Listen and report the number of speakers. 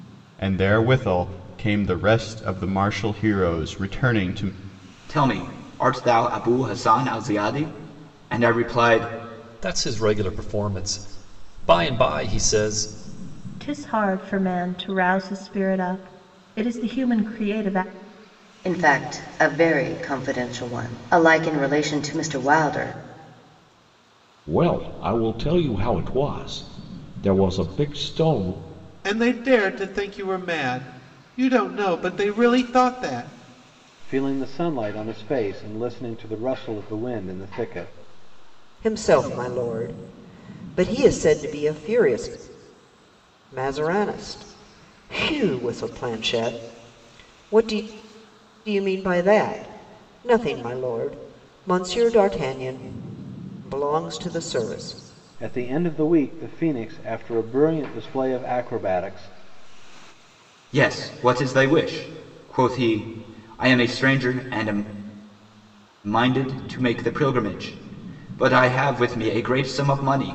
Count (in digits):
9